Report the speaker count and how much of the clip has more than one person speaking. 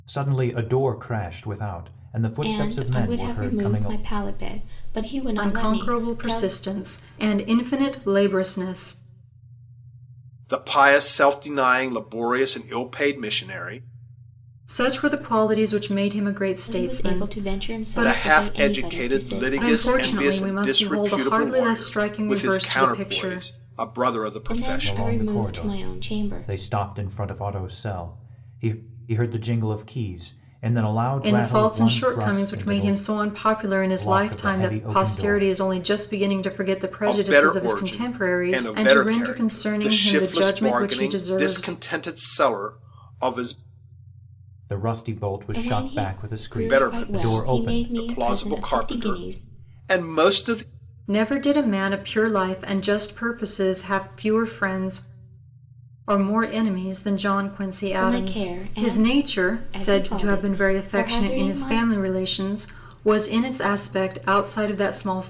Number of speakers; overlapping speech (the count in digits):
4, about 42%